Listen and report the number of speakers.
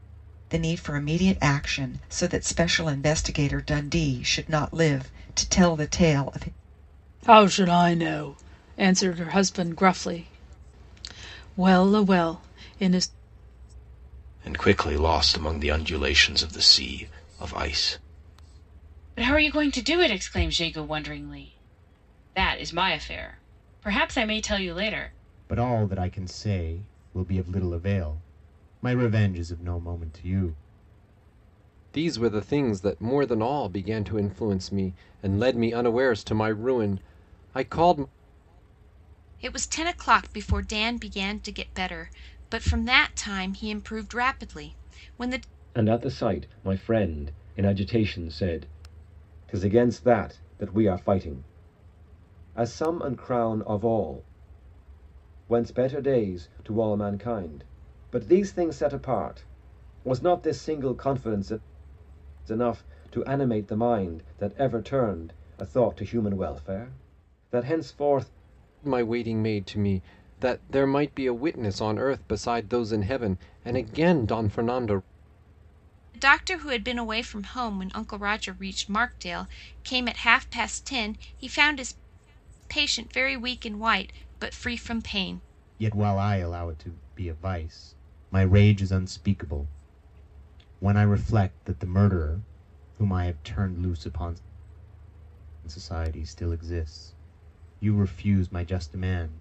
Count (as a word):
eight